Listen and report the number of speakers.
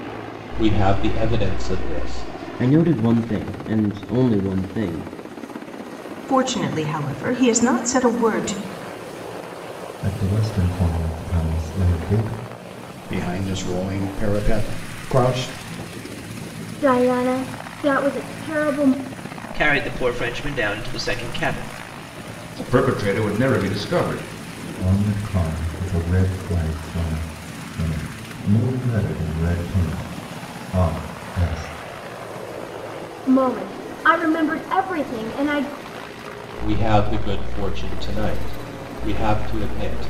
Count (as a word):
eight